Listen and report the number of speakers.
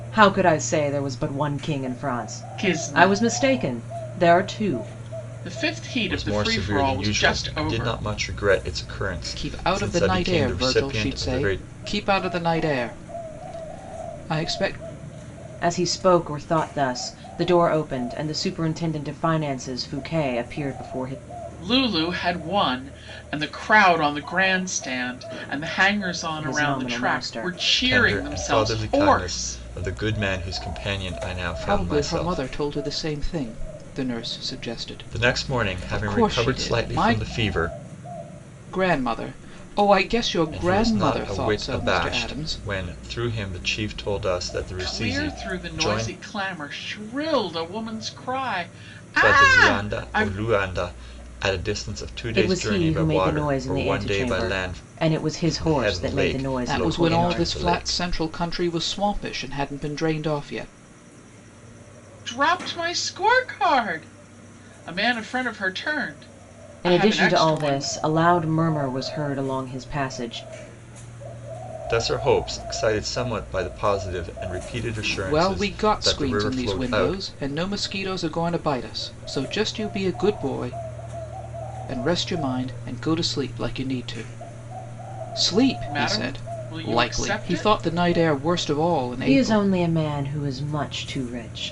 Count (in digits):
4